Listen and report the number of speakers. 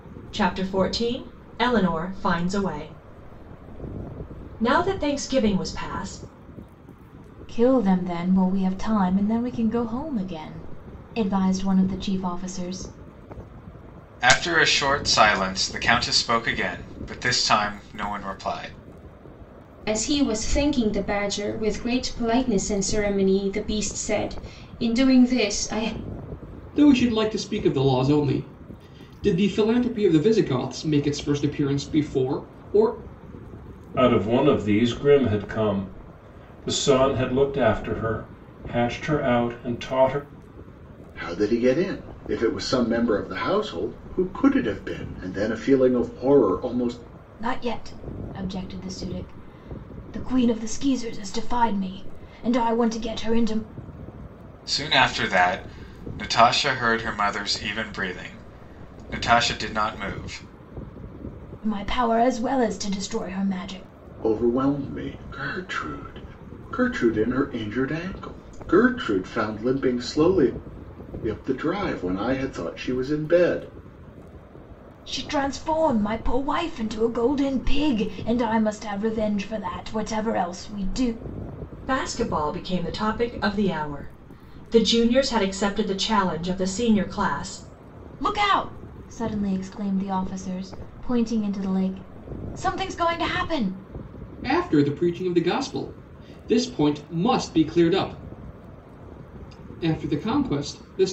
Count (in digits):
7